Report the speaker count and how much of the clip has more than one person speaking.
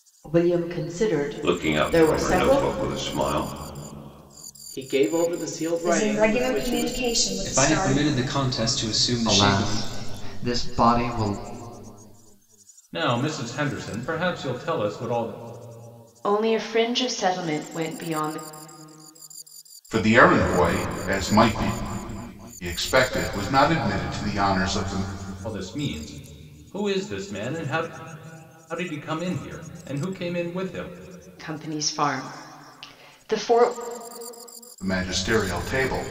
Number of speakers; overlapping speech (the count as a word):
nine, about 10%